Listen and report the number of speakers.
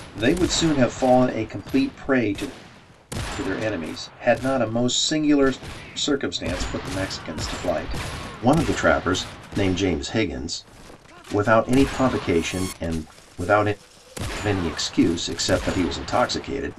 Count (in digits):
1